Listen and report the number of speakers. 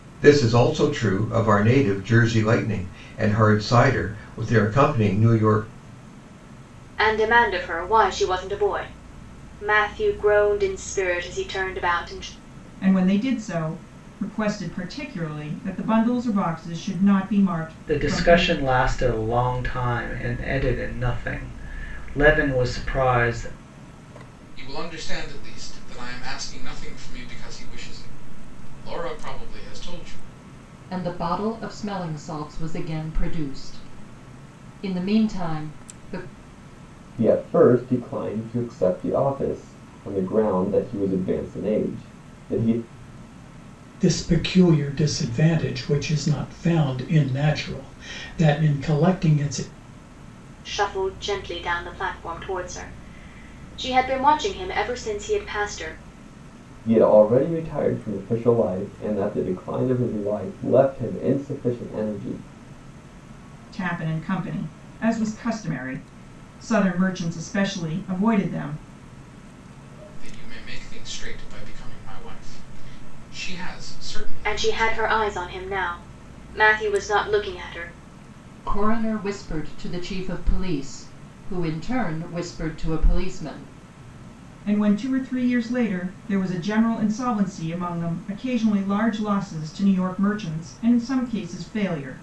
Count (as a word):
eight